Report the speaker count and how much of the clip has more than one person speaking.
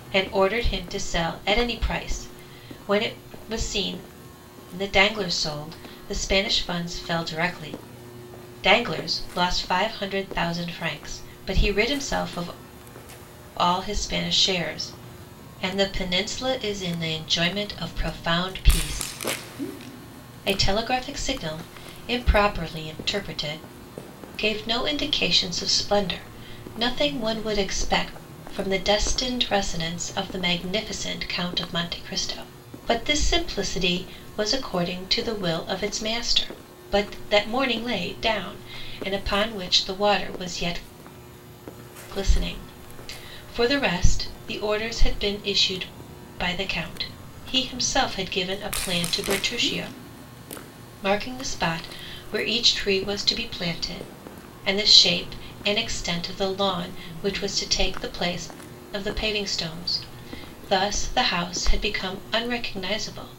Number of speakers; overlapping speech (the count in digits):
1, no overlap